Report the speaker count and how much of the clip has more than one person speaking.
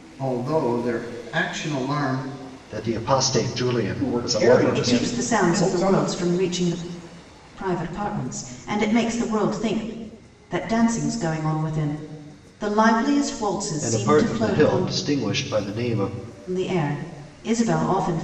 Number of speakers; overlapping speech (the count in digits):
4, about 18%